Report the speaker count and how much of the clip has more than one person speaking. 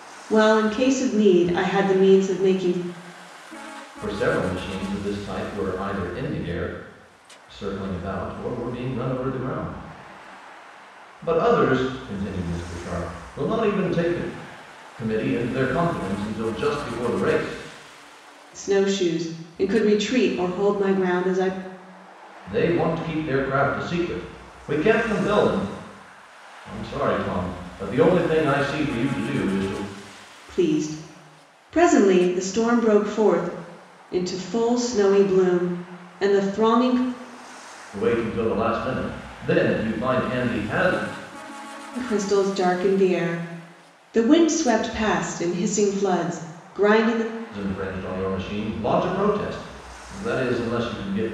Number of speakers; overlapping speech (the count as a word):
two, no overlap